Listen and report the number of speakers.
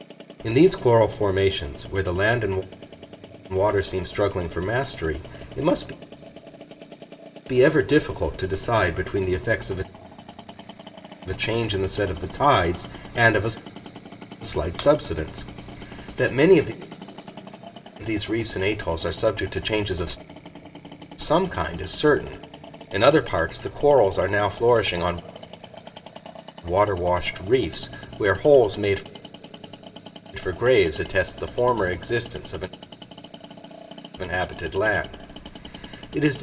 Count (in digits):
1